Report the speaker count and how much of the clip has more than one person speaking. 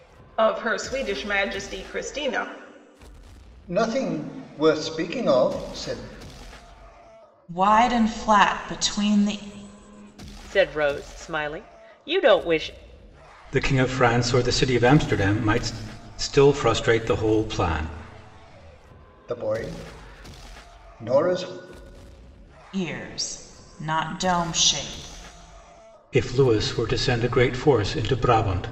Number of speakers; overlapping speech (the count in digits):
5, no overlap